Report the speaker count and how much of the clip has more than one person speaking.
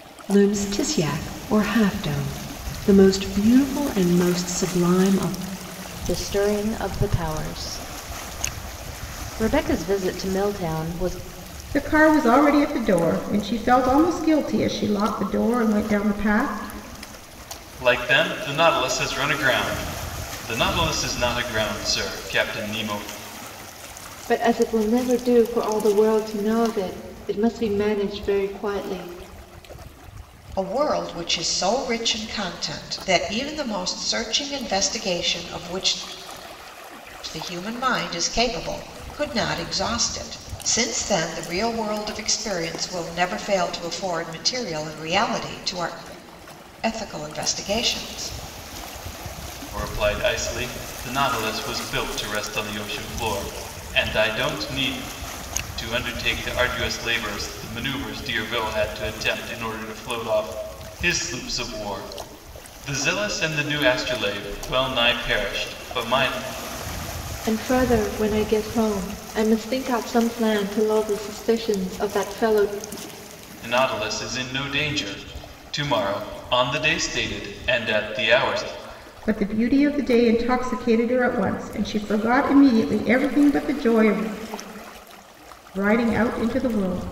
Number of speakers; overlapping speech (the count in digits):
6, no overlap